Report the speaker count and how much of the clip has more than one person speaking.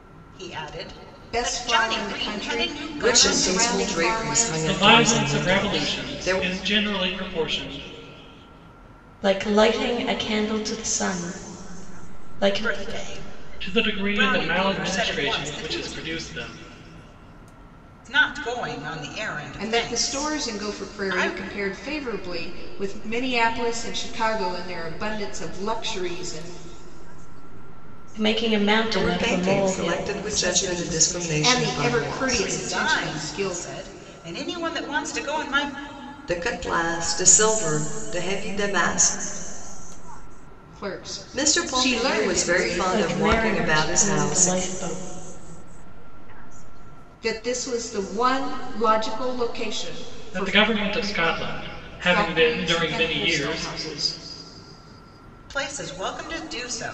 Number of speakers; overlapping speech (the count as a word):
six, about 58%